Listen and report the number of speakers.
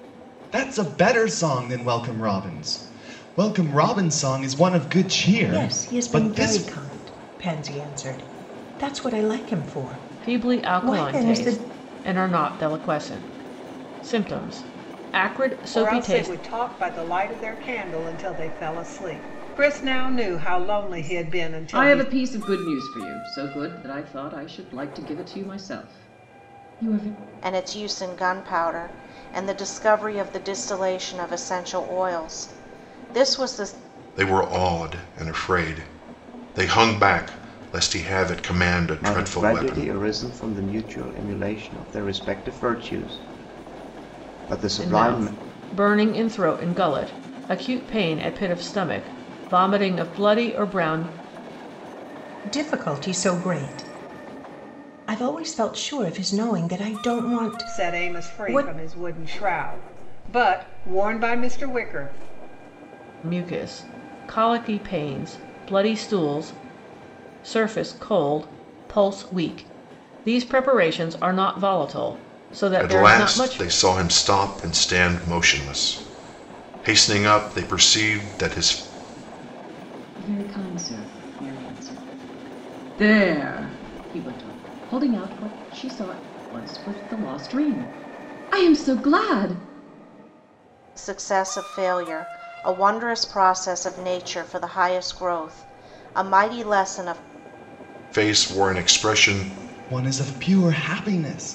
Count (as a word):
eight